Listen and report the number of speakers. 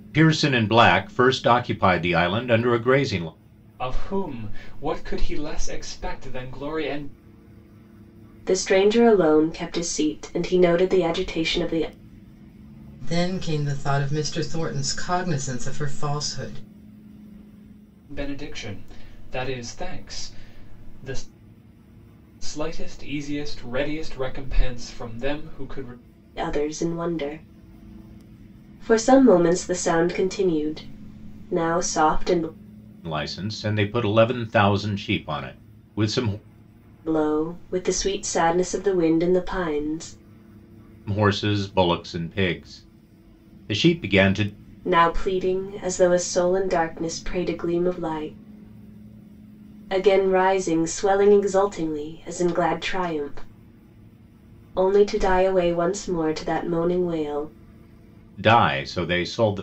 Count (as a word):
four